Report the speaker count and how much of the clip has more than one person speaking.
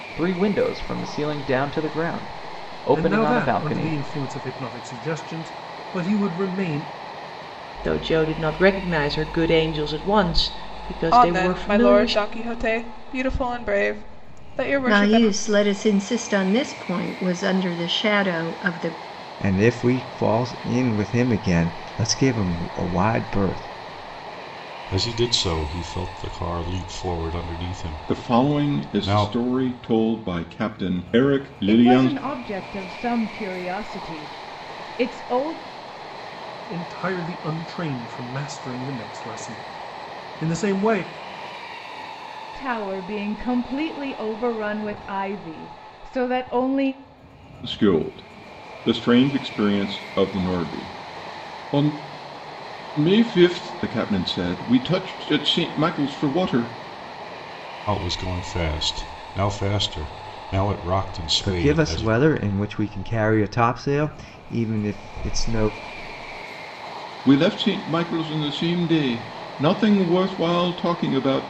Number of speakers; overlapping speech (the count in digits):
9, about 7%